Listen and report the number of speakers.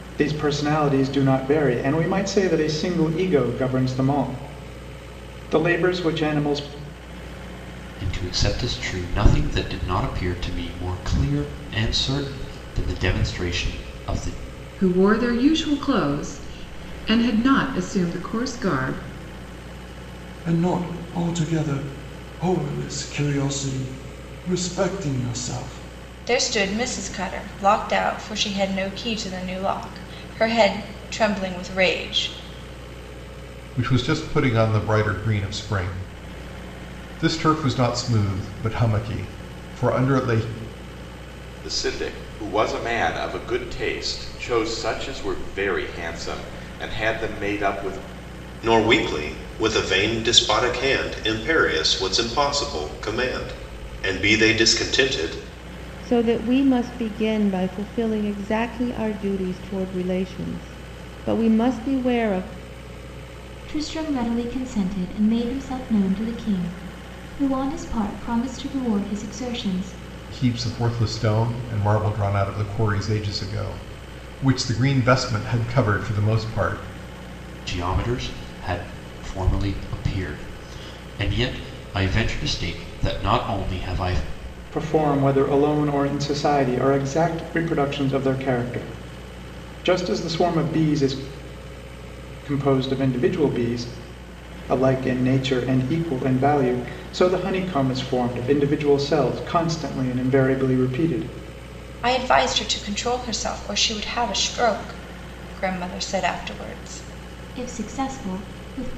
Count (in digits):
10